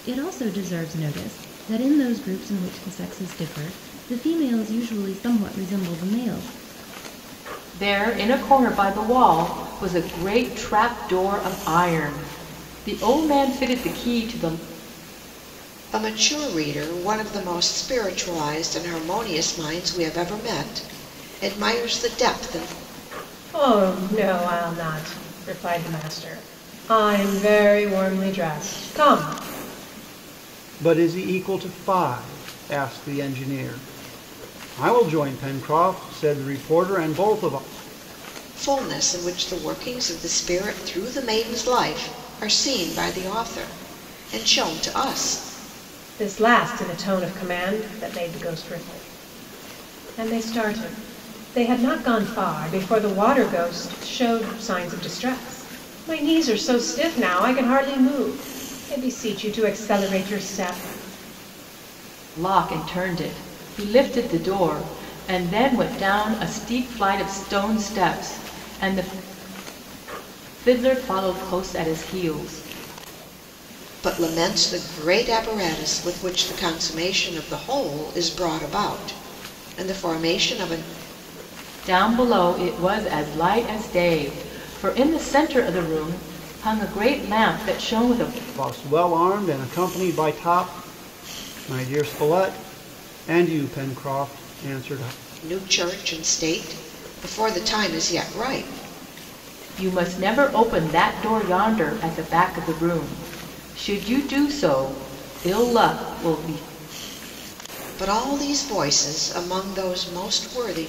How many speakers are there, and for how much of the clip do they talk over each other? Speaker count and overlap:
5, no overlap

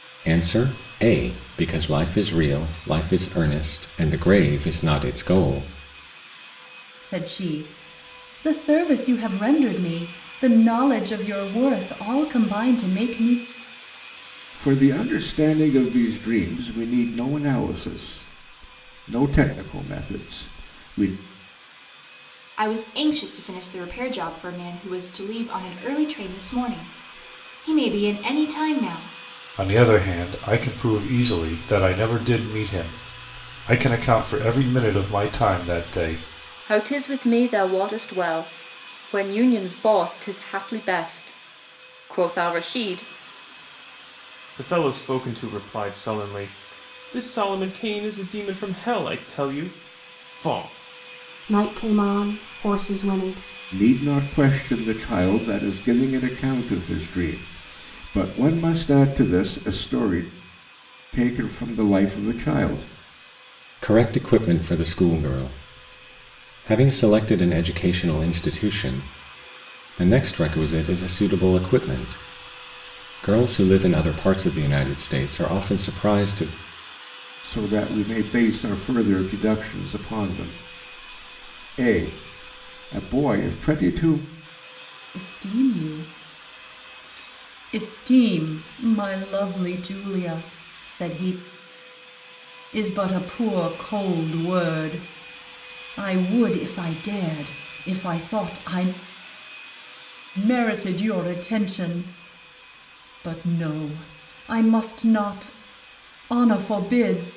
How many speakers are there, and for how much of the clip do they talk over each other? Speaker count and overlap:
8, no overlap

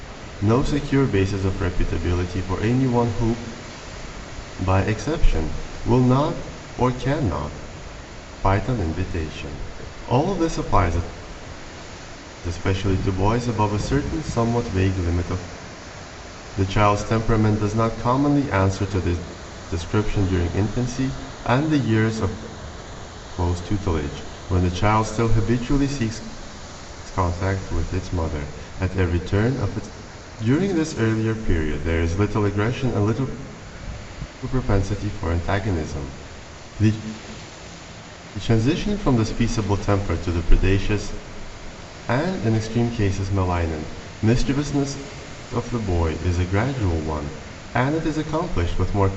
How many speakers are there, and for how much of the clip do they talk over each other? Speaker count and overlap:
1, no overlap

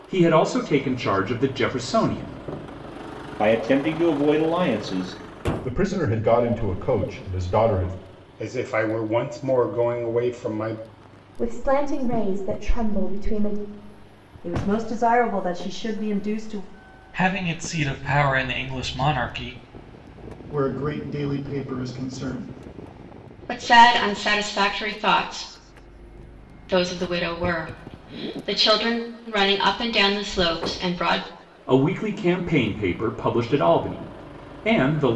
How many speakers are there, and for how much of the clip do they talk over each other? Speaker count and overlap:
9, no overlap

